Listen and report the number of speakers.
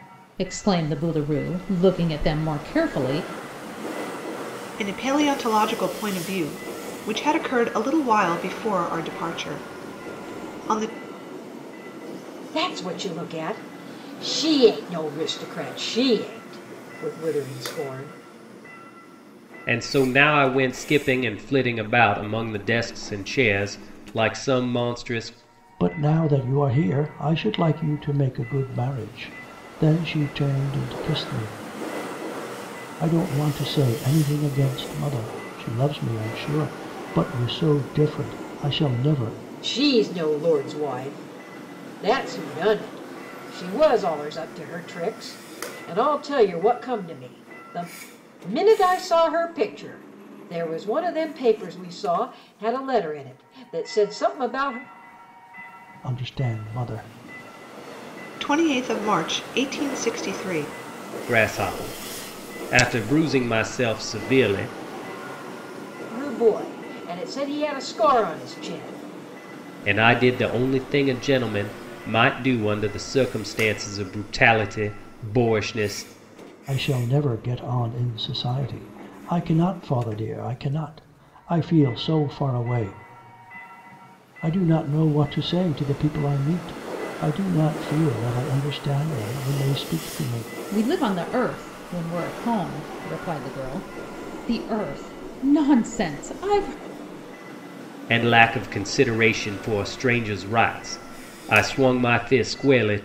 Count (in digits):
5